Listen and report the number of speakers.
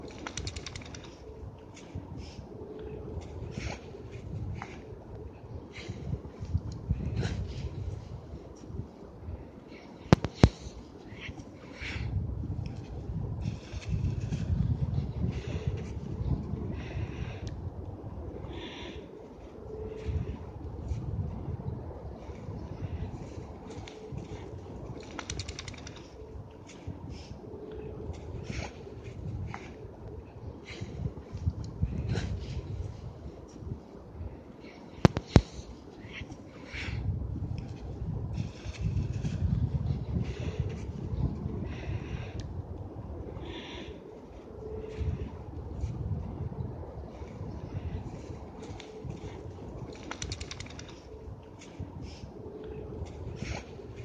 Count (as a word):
zero